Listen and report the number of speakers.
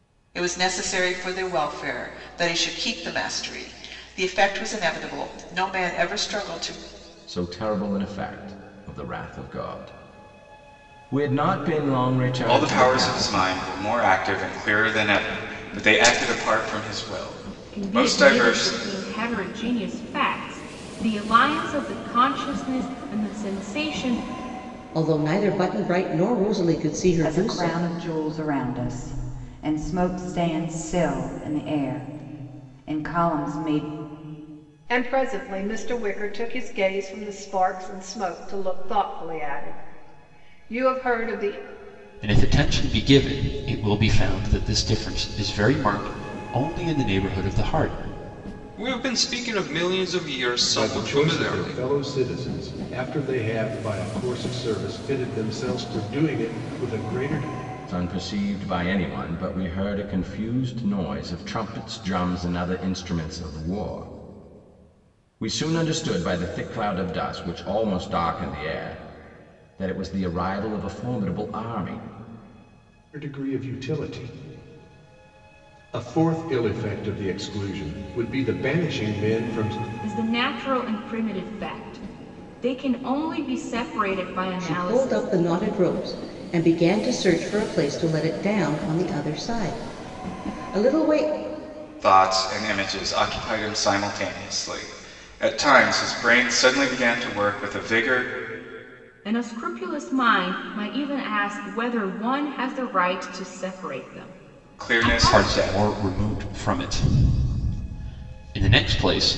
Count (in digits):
10